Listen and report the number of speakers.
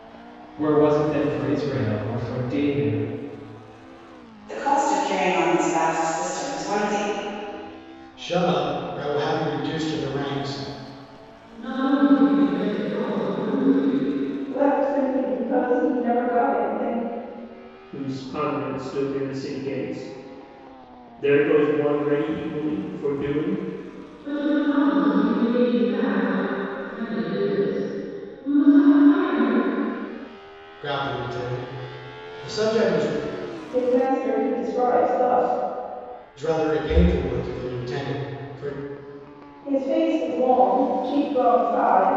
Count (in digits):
6